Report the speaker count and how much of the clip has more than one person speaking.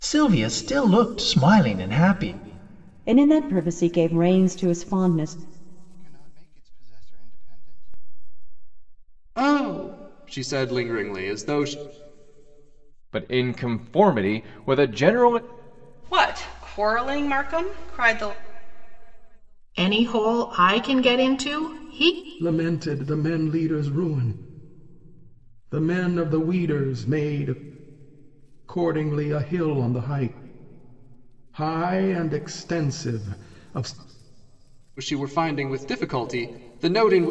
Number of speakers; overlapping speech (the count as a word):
eight, no overlap